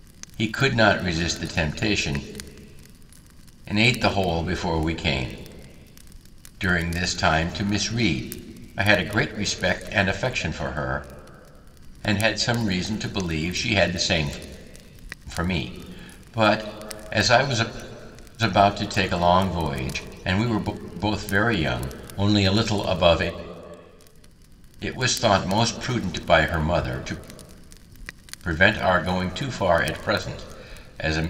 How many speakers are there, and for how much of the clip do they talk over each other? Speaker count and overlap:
one, no overlap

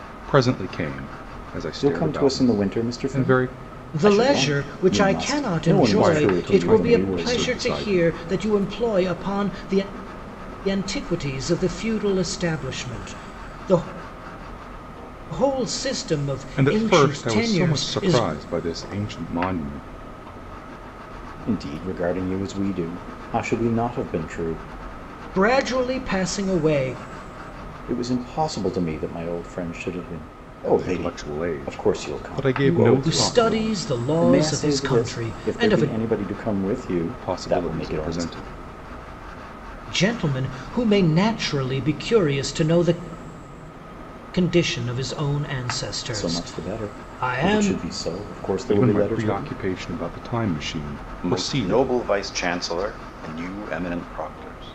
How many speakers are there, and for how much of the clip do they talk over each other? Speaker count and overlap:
three, about 31%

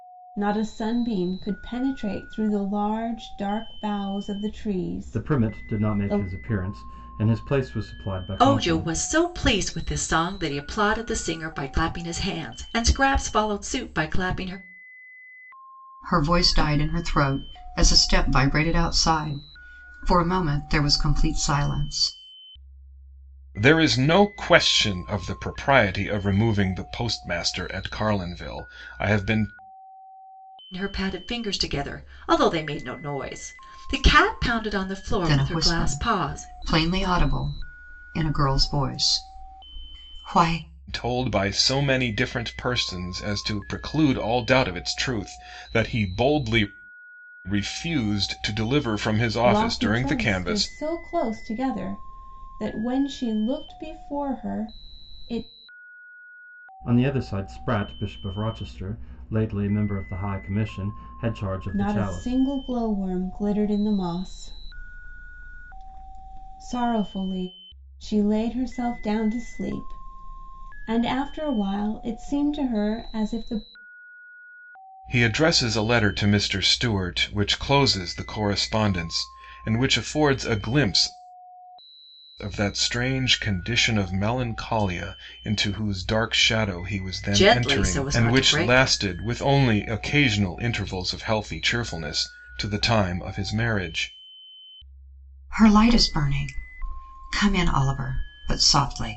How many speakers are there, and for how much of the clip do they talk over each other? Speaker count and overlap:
five, about 7%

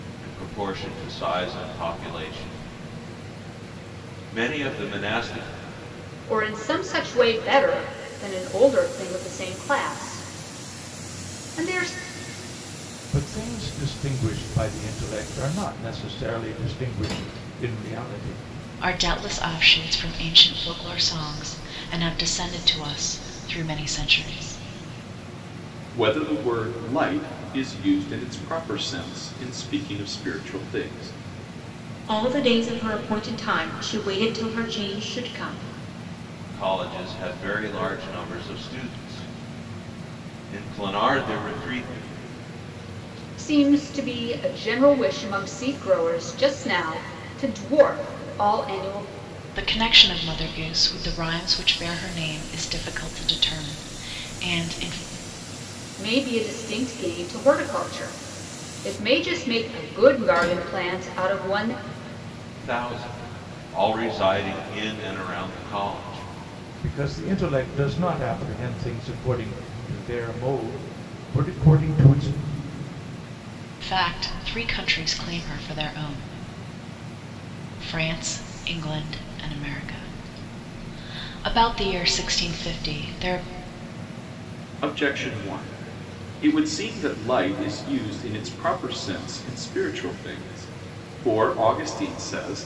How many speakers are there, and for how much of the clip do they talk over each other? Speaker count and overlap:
six, no overlap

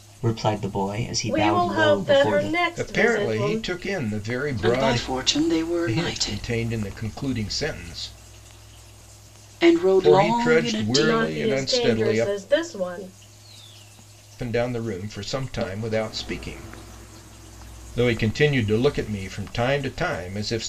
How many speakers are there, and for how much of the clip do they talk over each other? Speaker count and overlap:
four, about 28%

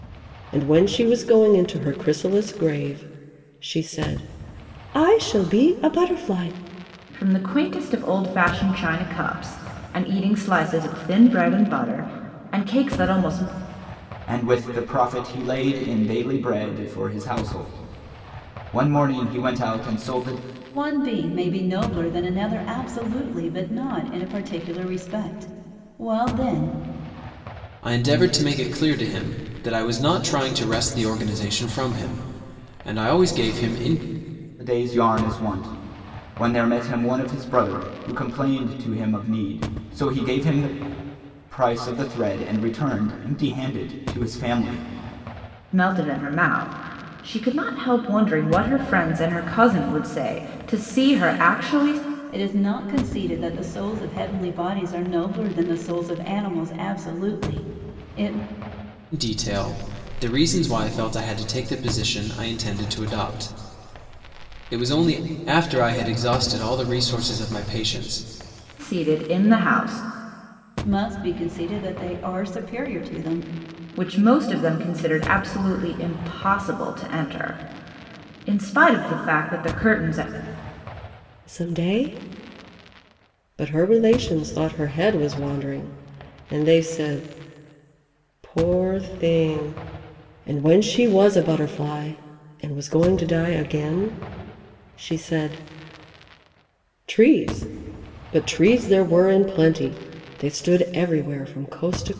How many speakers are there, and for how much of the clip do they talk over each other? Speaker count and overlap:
five, no overlap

